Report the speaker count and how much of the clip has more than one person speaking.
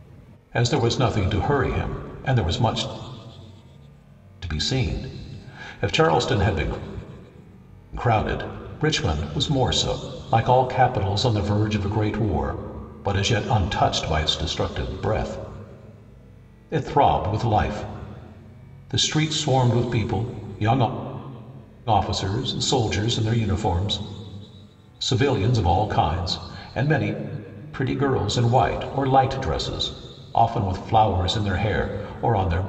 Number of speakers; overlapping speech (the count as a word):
one, no overlap